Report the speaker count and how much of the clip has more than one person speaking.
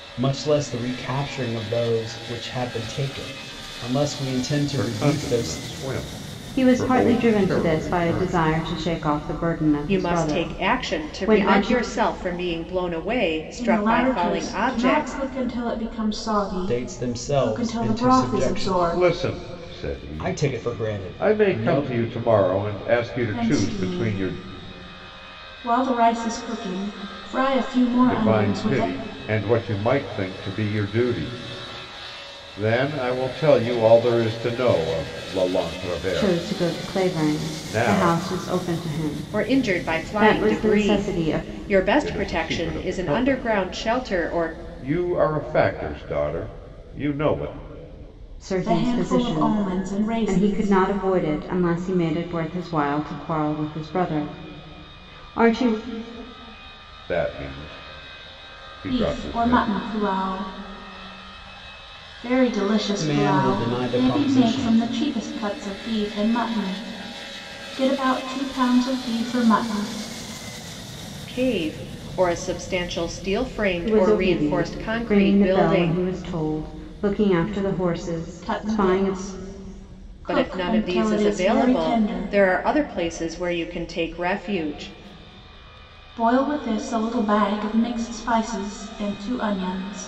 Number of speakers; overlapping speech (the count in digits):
5, about 34%